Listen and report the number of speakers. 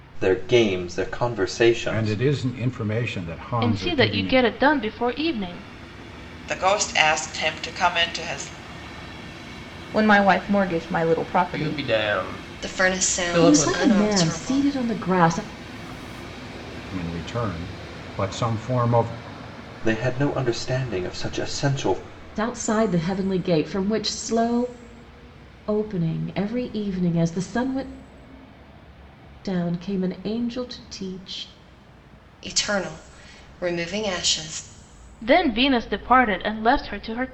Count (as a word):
eight